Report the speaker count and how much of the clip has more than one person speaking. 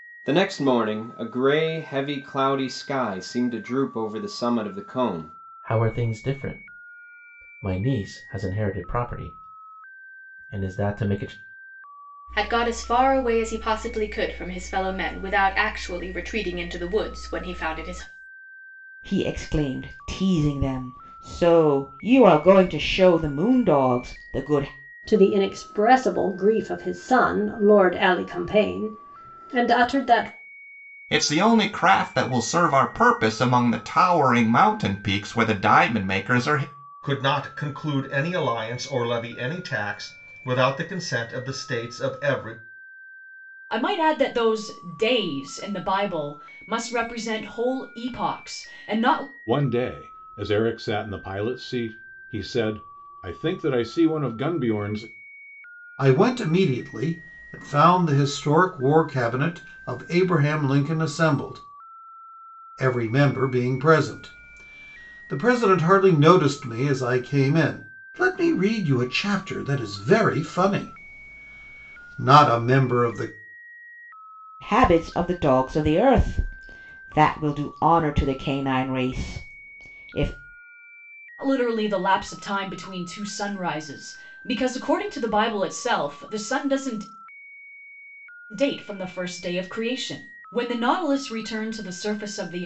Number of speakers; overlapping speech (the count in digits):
10, no overlap